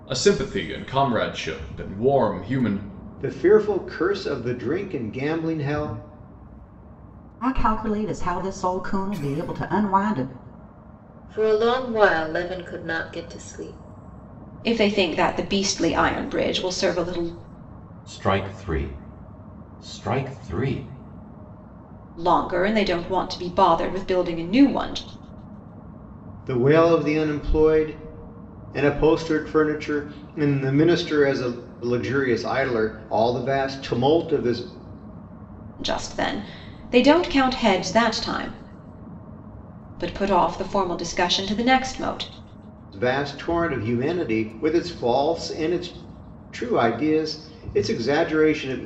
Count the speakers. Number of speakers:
6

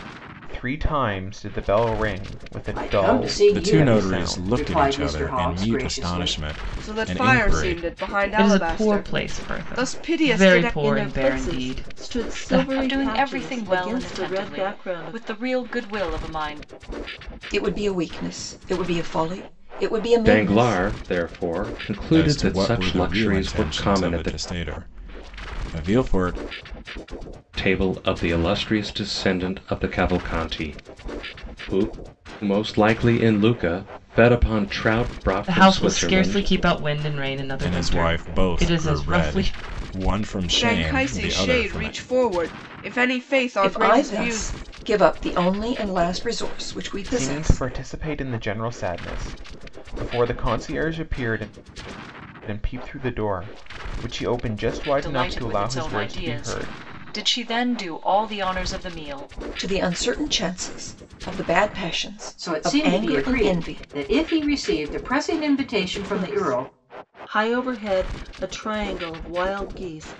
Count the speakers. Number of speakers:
9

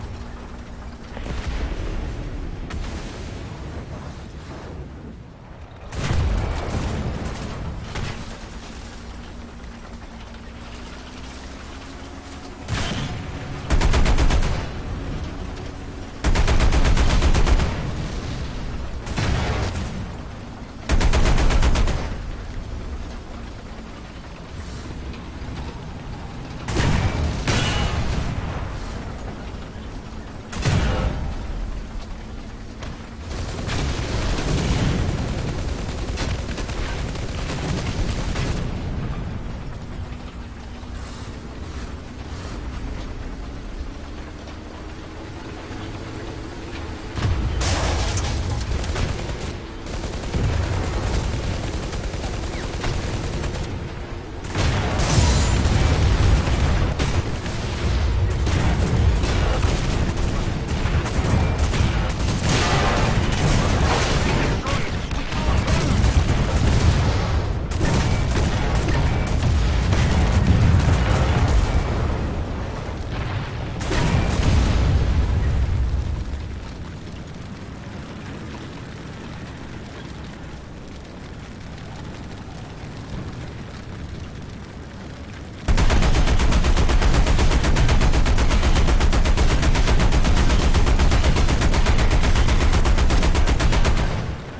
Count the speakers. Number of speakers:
0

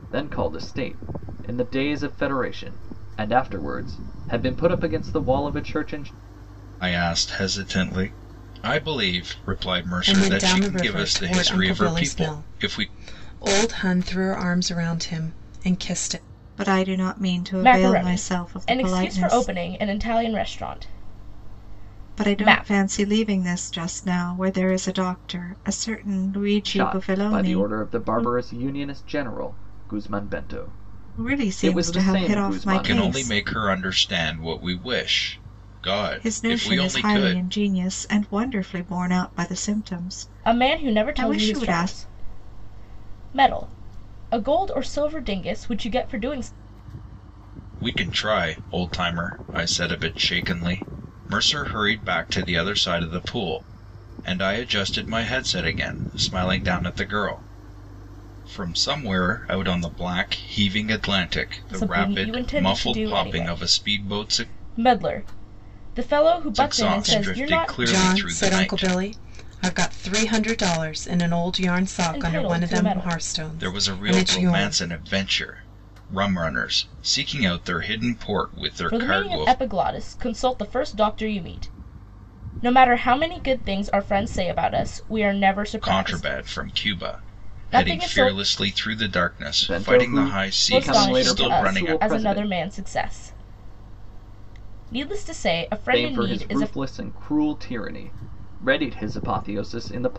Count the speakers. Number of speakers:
5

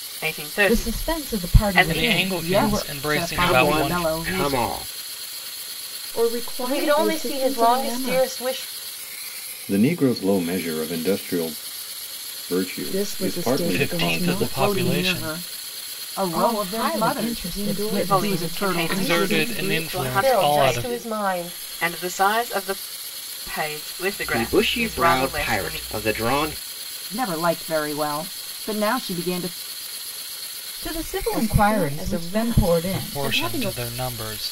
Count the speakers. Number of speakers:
8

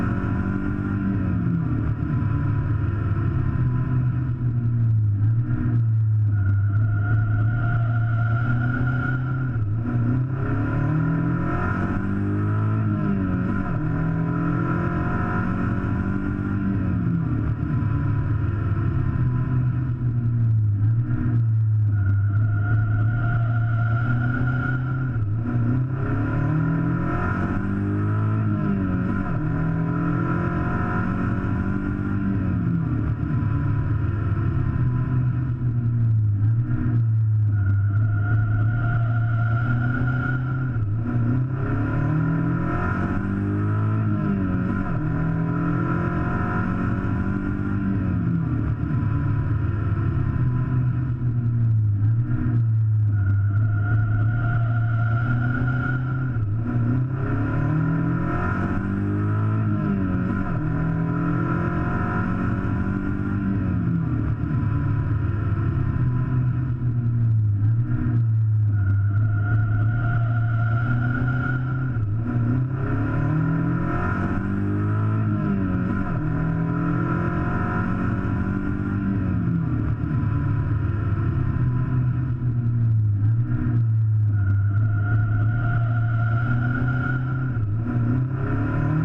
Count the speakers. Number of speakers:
0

